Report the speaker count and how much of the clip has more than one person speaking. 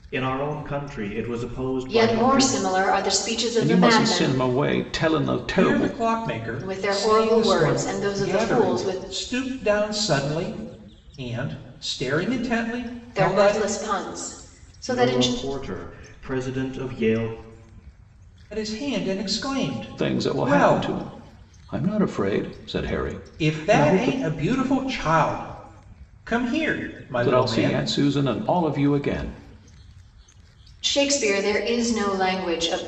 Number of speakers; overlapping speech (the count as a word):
four, about 23%